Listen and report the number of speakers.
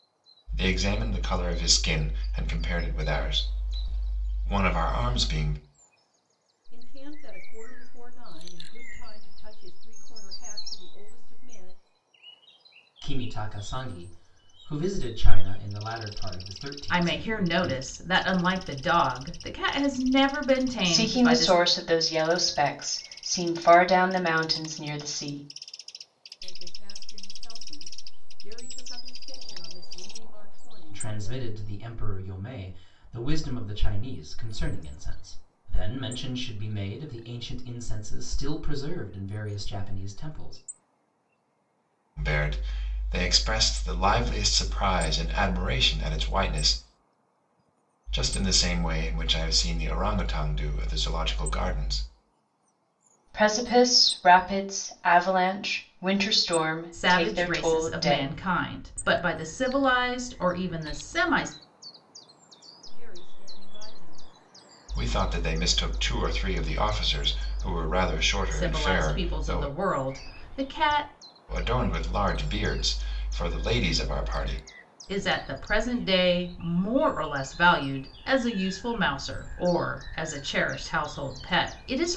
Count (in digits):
5